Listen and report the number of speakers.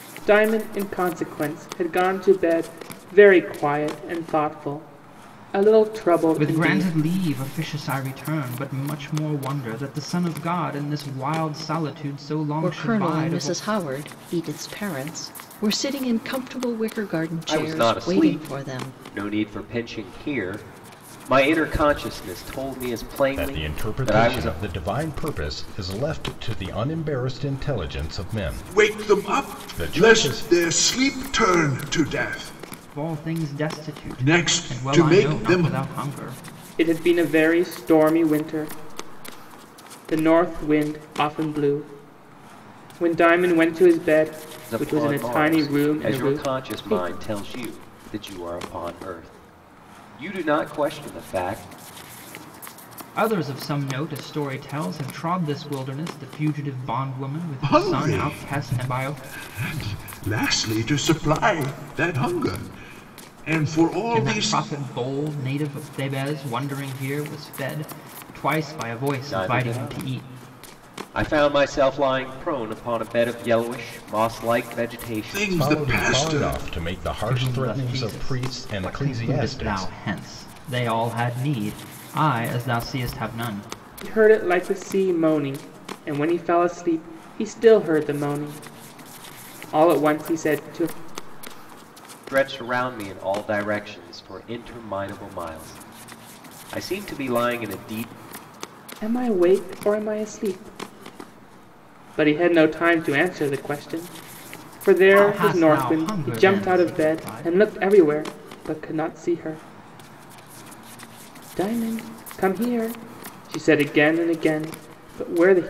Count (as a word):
six